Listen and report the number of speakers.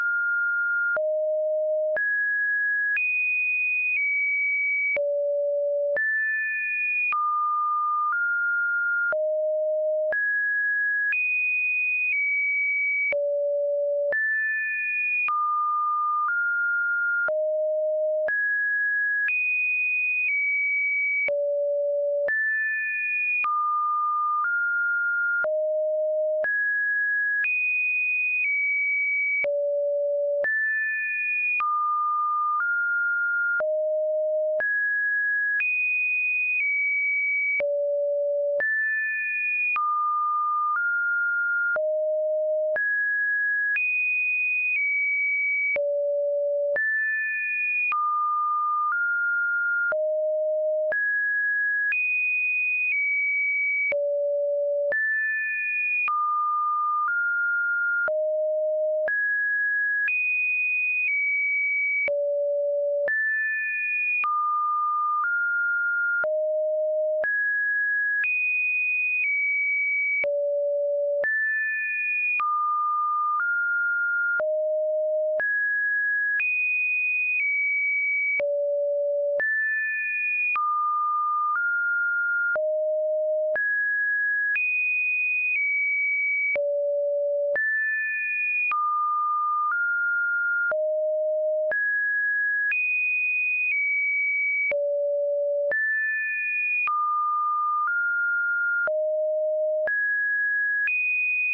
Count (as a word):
zero